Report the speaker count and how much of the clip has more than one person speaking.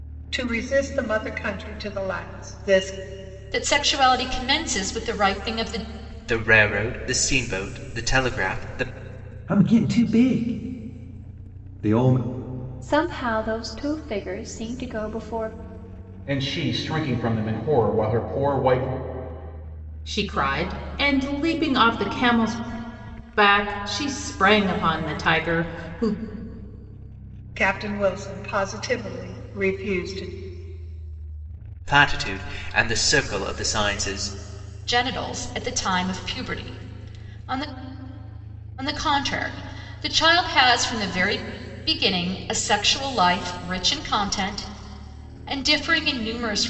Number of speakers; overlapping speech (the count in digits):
7, no overlap